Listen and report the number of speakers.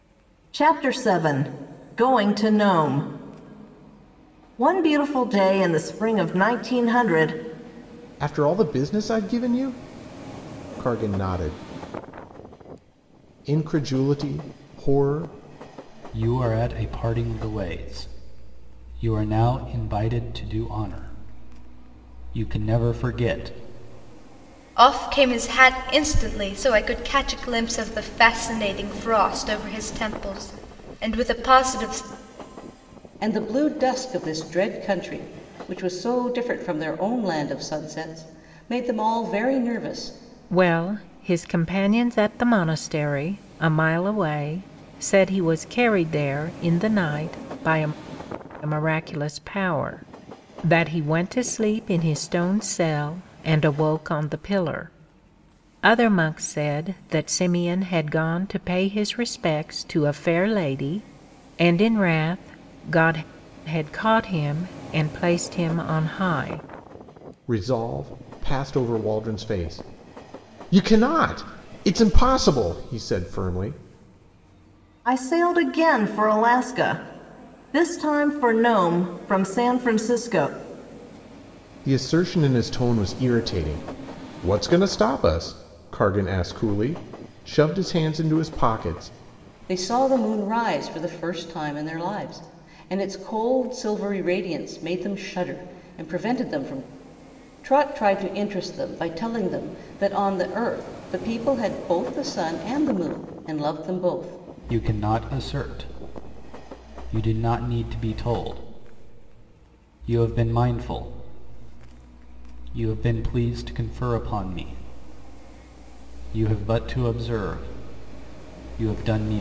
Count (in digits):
6